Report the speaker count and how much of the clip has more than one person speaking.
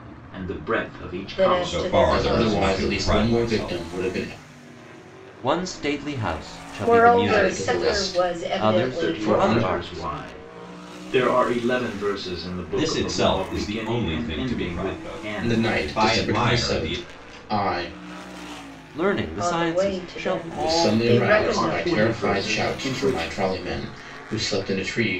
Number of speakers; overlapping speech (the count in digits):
5, about 56%